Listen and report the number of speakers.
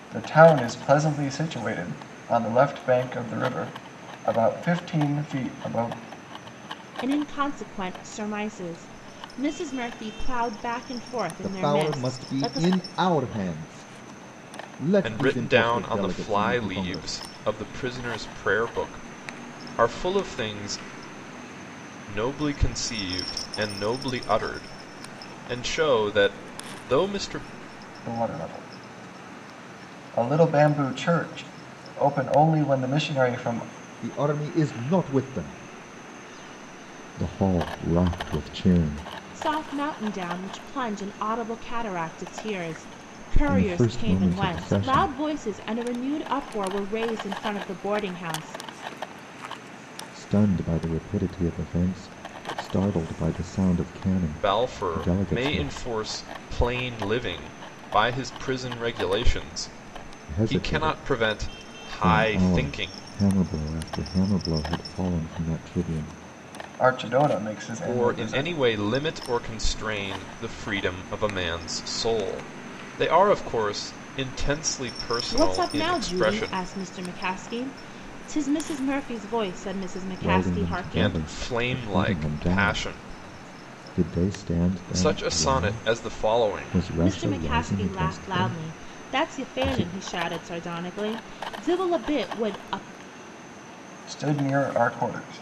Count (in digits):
4